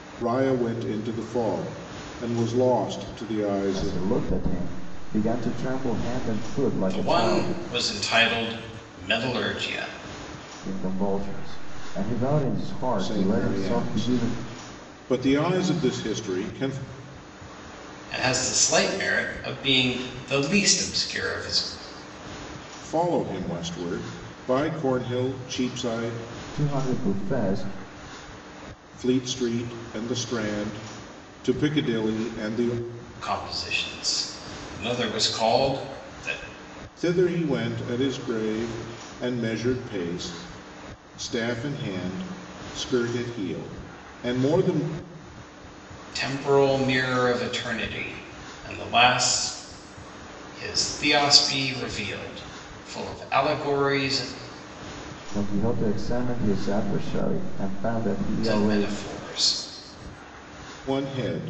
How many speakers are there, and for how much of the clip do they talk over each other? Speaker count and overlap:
3, about 5%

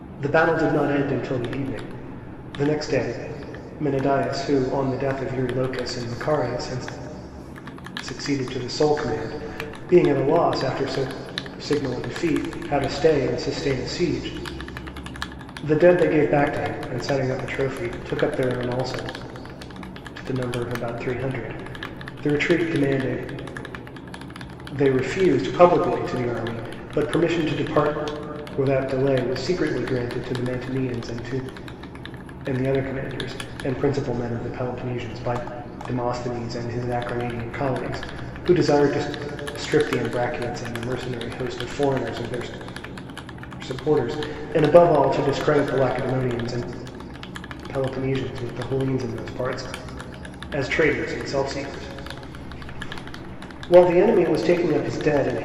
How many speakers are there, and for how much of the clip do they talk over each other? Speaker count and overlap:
1, no overlap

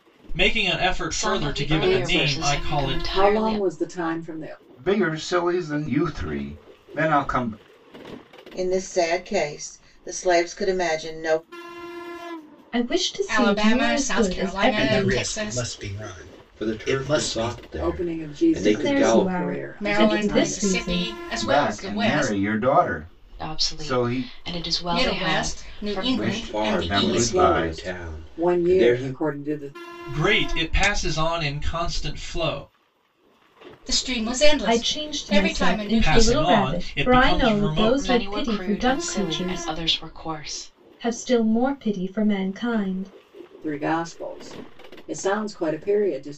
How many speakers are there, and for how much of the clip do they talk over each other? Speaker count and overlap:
9, about 44%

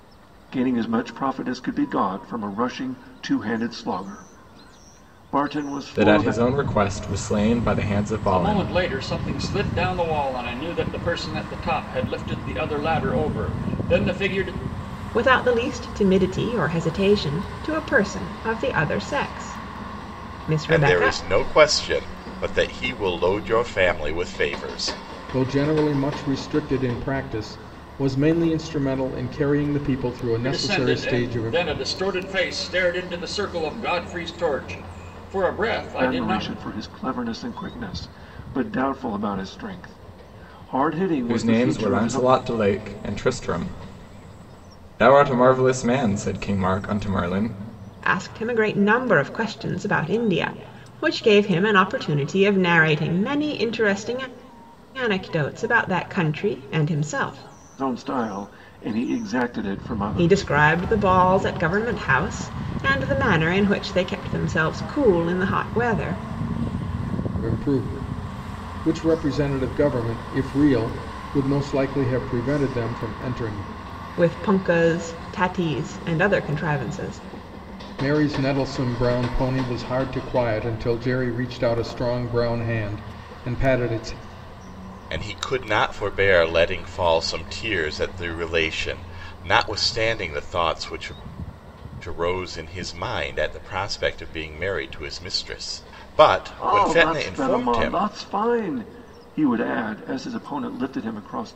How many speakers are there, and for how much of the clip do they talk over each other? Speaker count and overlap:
6, about 6%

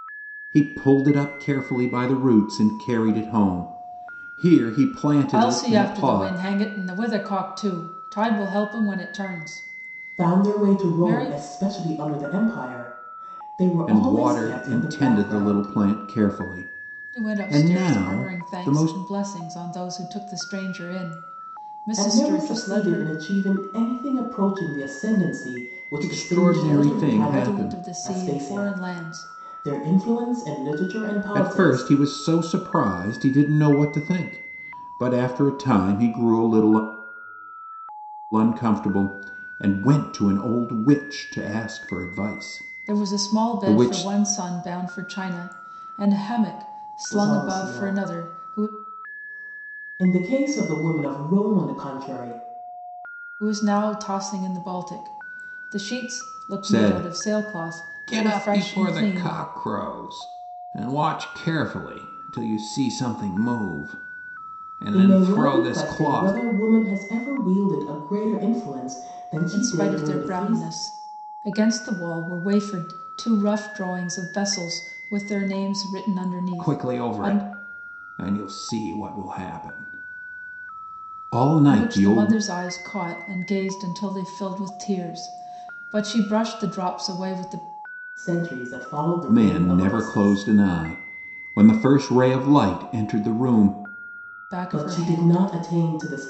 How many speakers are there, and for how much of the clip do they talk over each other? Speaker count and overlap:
3, about 24%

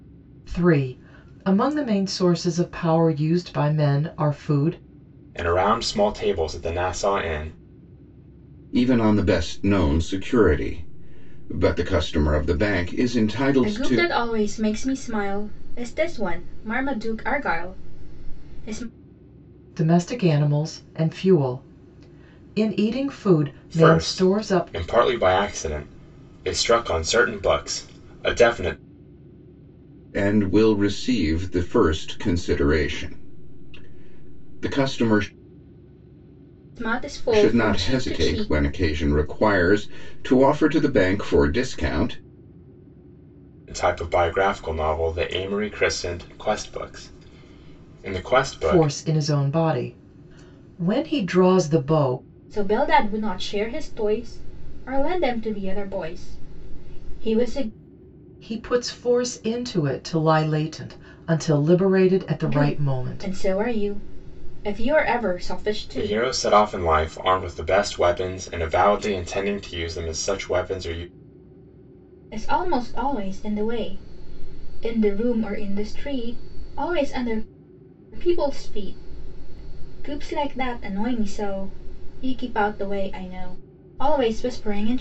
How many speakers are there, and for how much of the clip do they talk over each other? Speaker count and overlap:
4, about 5%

